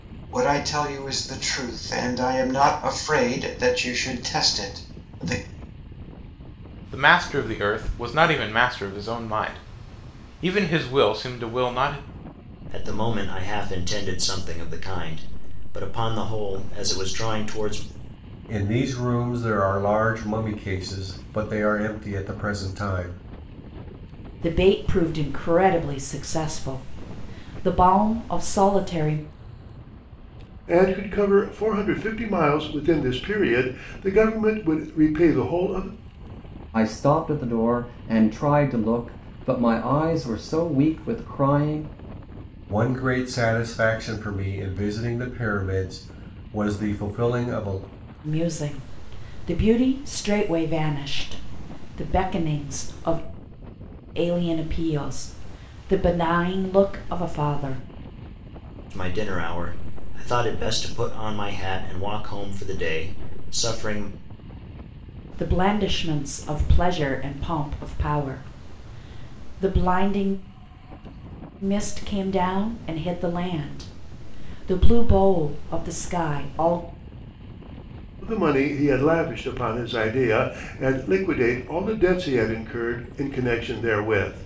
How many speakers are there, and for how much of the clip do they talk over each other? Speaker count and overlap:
7, no overlap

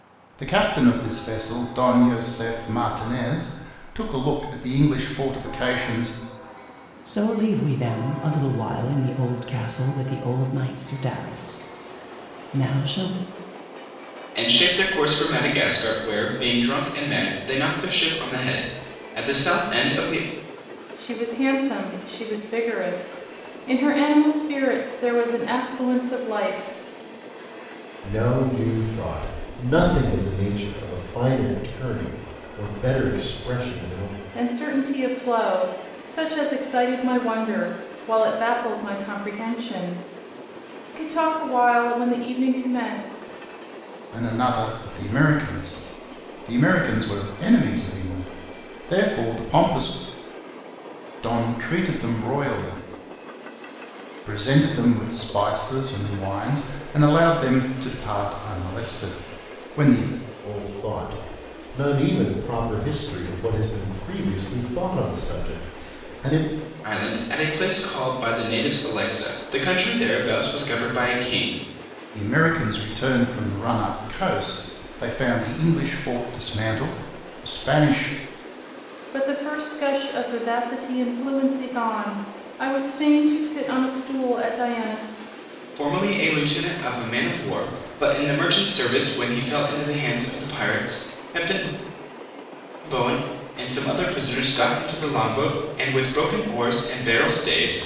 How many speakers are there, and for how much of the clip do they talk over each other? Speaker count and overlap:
5, no overlap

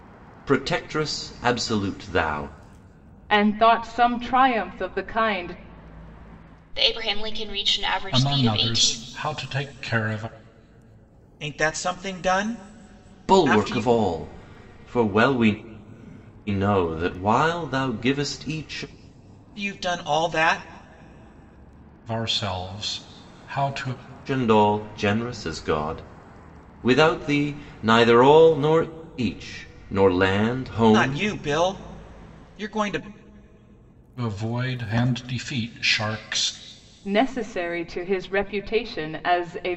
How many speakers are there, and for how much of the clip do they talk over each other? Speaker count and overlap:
5, about 5%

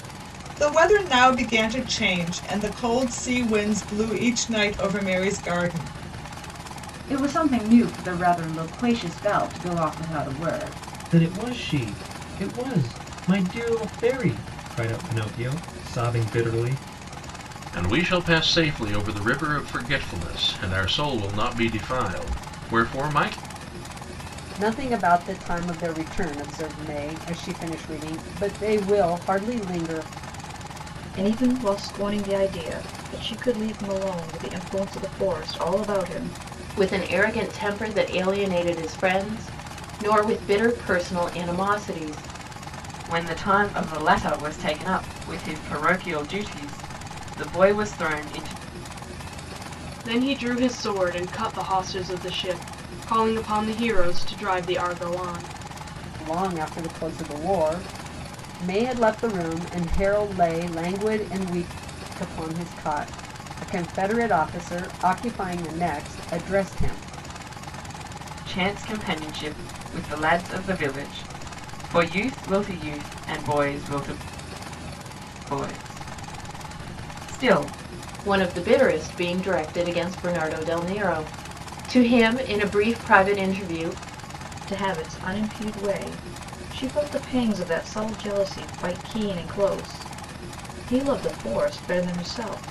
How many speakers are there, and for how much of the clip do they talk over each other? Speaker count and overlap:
9, no overlap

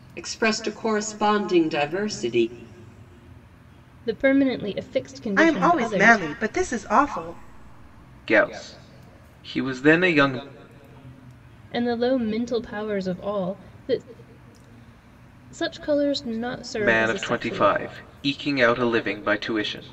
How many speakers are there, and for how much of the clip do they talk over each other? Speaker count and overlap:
4, about 9%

